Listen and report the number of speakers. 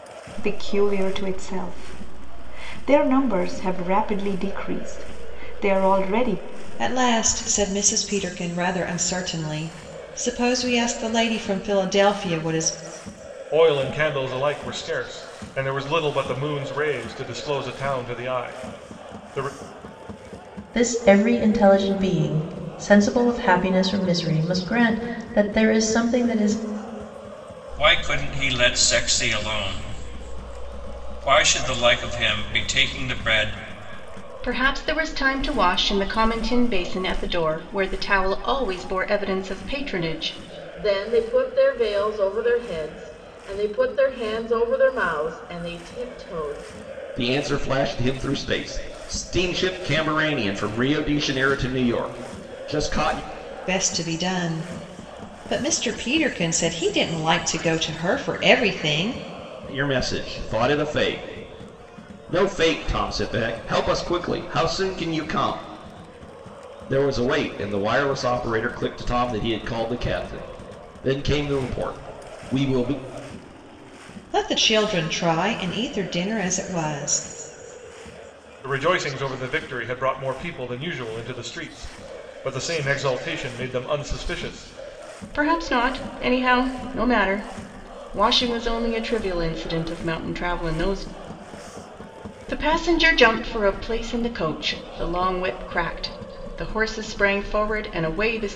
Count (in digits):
8